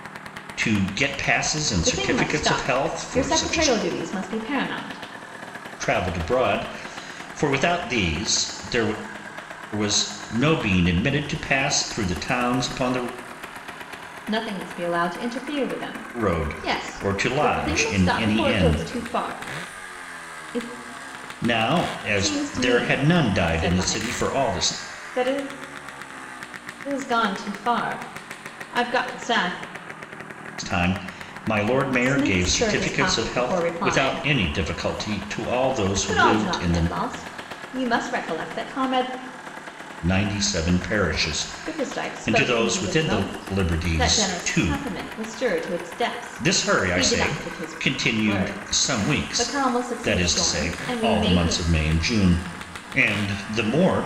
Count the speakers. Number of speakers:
two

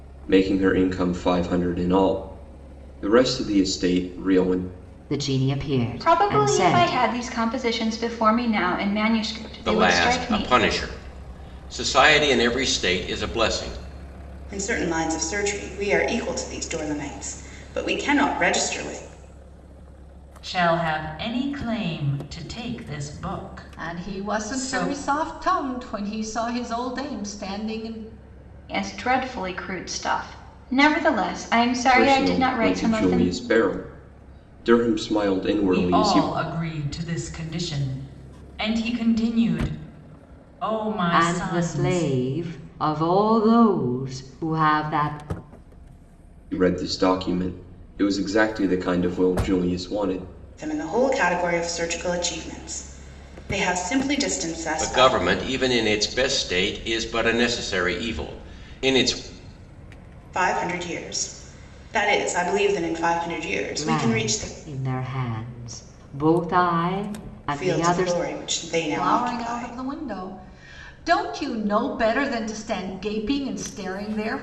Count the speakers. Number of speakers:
seven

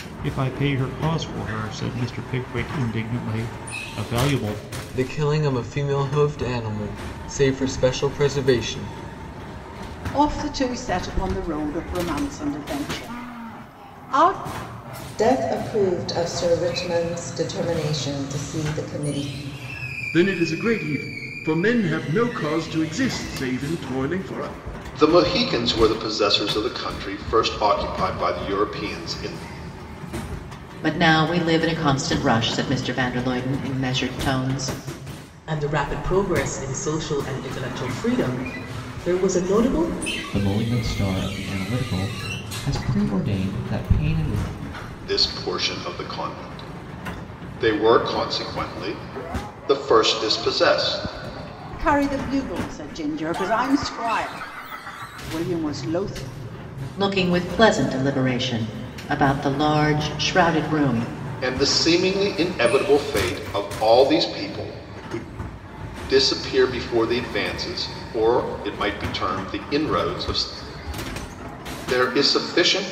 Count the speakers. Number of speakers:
nine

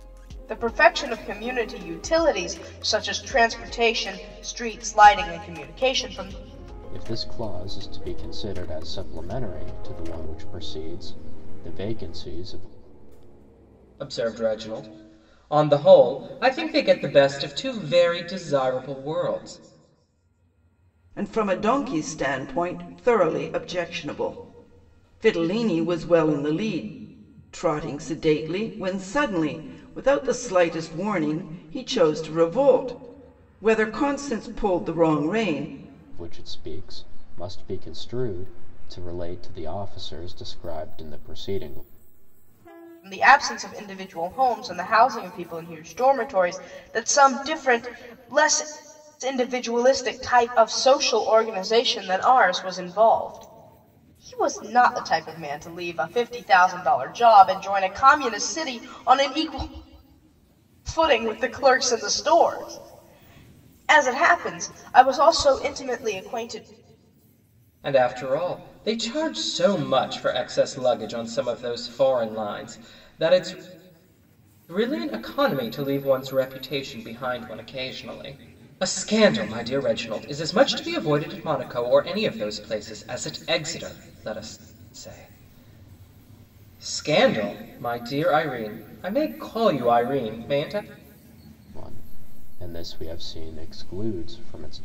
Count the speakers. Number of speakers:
four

